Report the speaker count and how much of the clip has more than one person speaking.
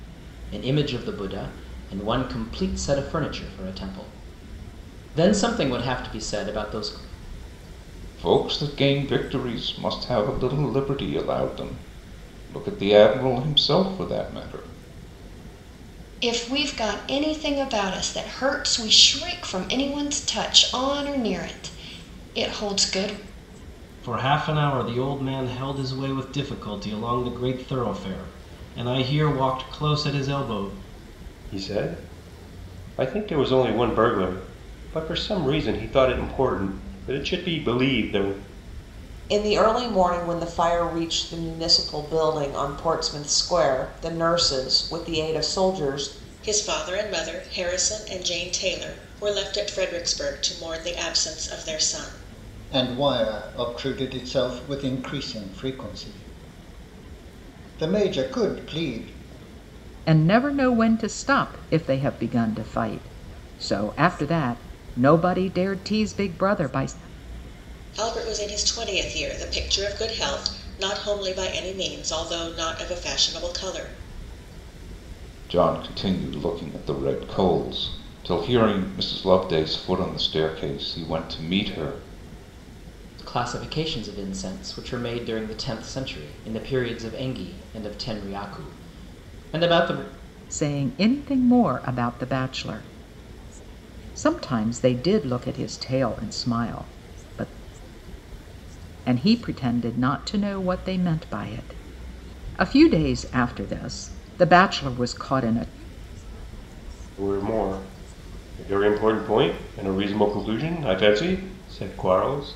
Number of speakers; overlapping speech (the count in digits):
9, no overlap